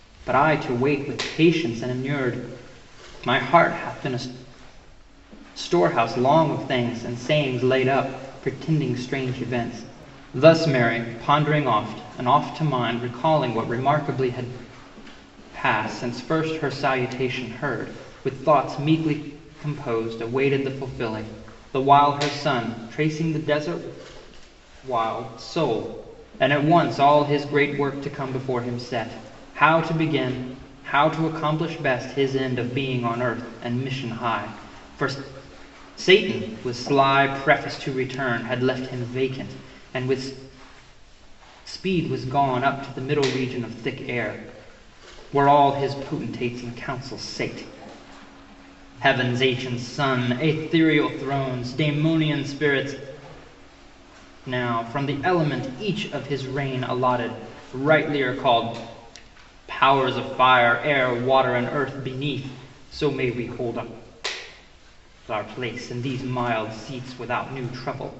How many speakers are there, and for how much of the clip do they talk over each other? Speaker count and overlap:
1, no overlap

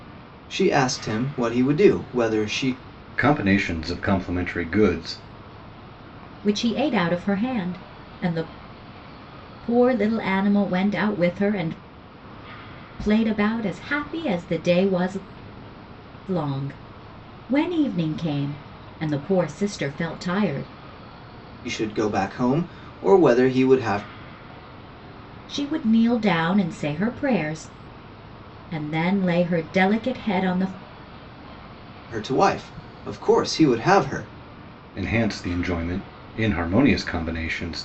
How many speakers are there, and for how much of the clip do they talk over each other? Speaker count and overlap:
3, no overlap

